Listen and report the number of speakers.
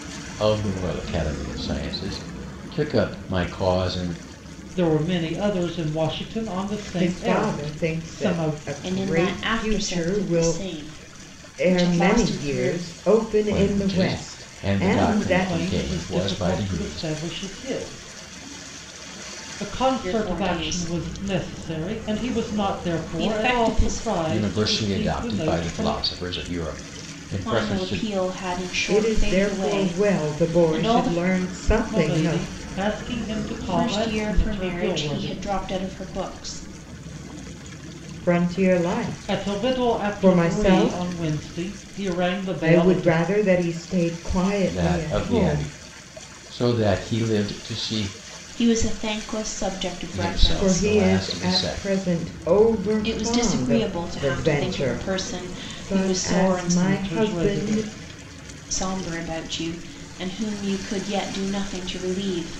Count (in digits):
4